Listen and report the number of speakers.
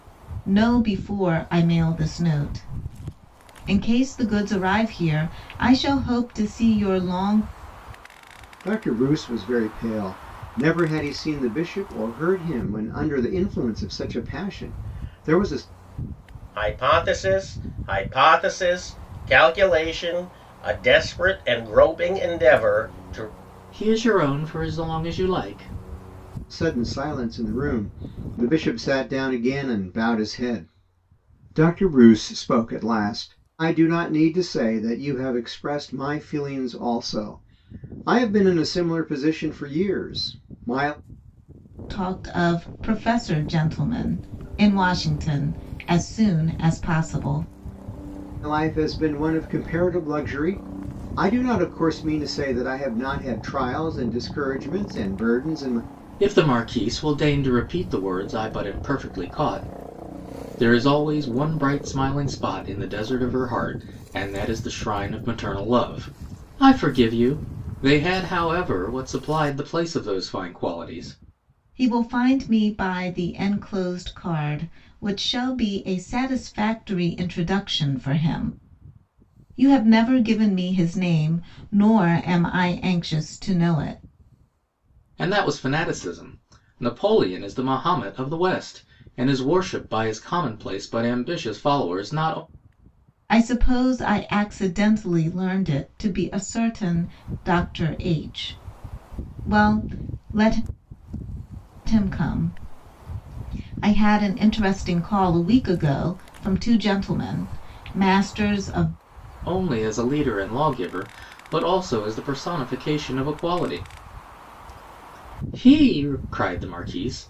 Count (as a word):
four